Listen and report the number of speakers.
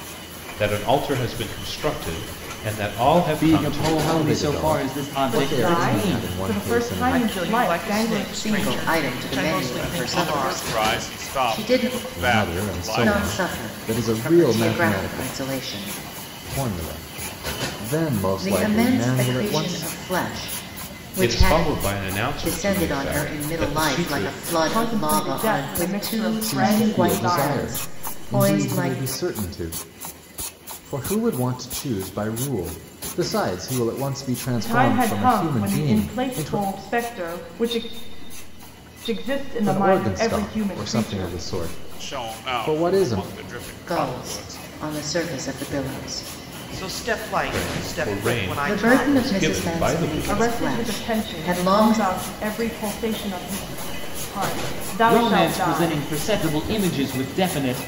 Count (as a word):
seven